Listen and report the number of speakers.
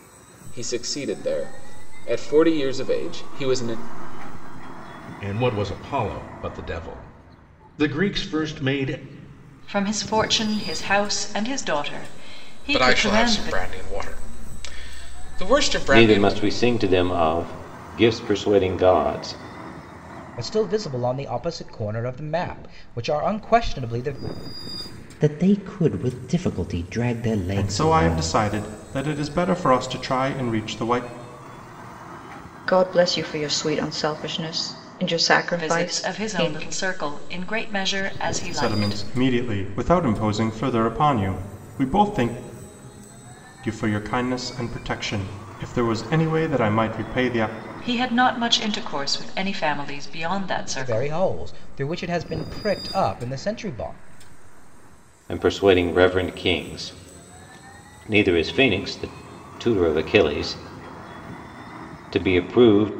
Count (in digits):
9